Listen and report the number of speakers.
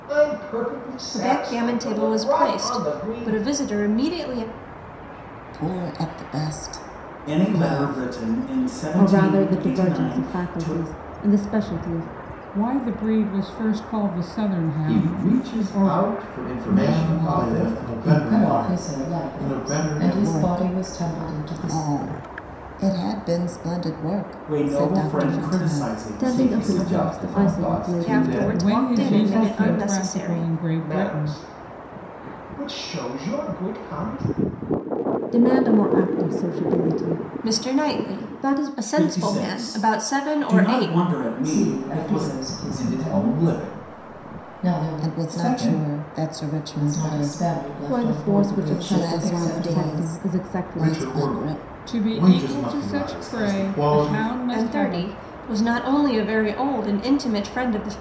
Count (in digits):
9